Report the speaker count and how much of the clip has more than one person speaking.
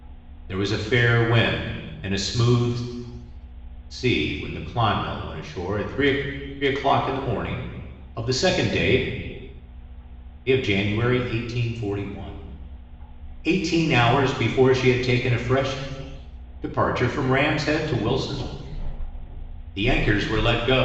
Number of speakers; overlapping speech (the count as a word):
one, no overlap